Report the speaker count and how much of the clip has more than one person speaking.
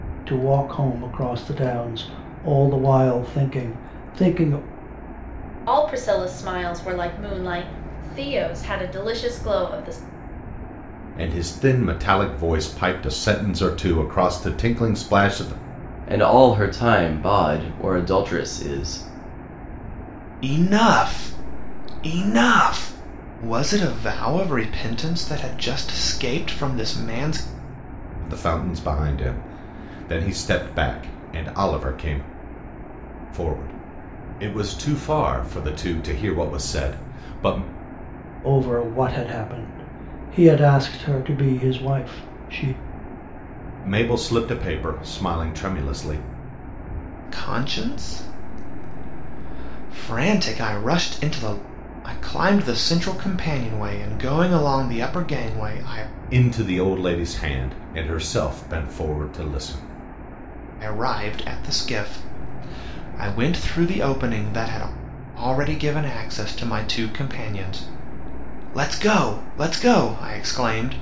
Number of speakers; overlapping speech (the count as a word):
five, no overlap